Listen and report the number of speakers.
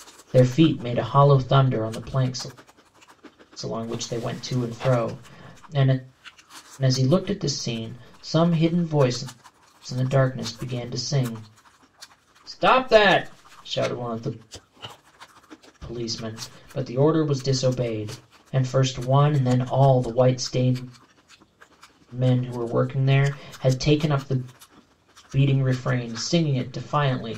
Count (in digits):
1